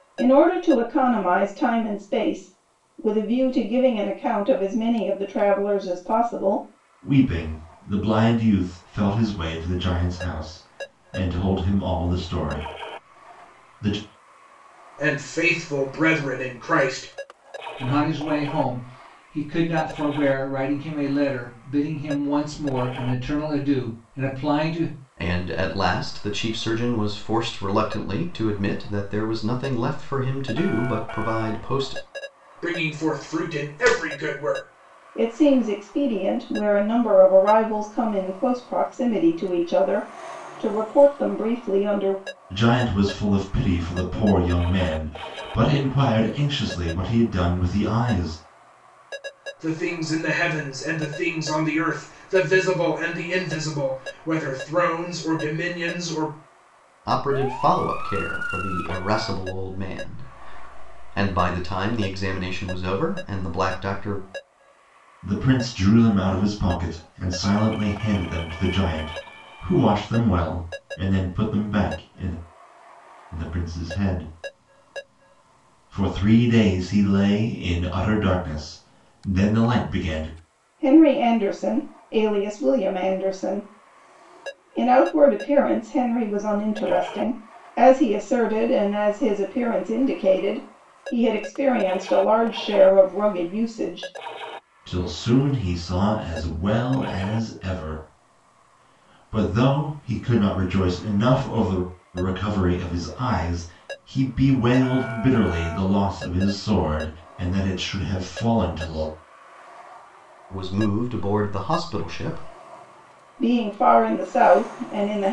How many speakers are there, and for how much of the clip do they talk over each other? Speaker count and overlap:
5, no overlap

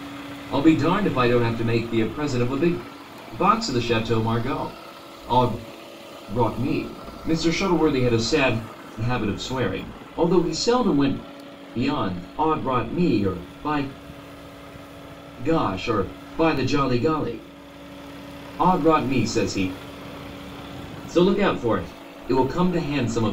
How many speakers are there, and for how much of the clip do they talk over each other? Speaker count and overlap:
1, no overlap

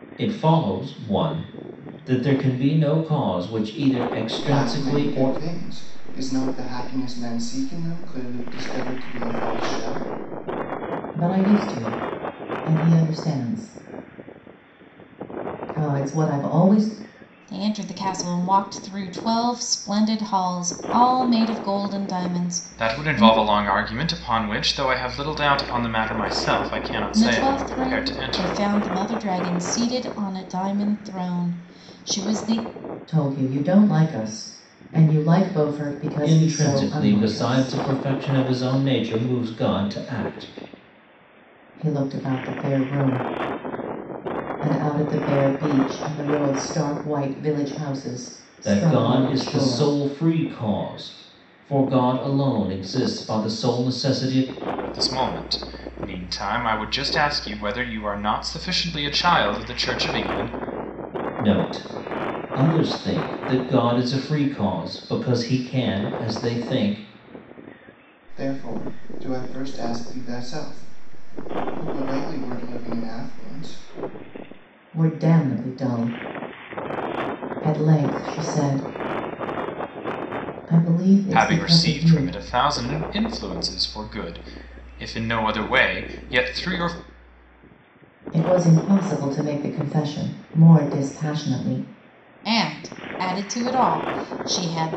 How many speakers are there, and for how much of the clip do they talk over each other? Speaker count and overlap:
5, about 7%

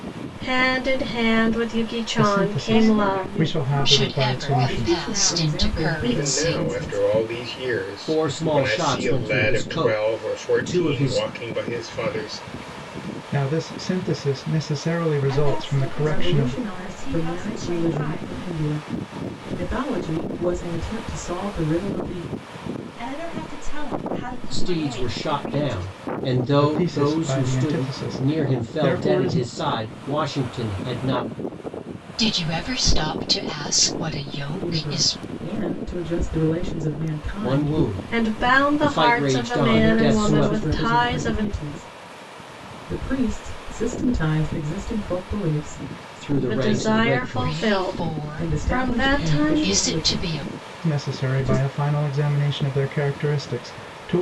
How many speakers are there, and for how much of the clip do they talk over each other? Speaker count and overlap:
7, about 45%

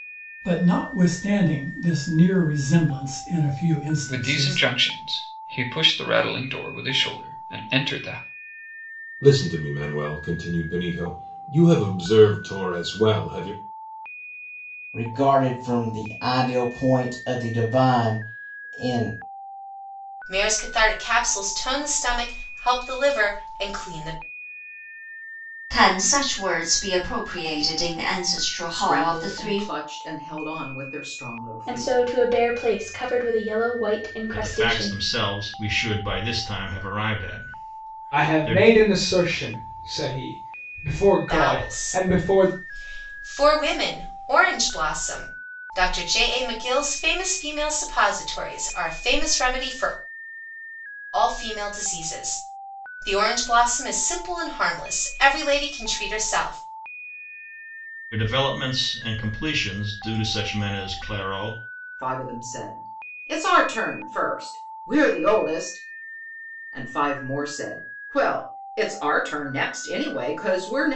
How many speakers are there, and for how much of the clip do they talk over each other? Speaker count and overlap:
10, about 6%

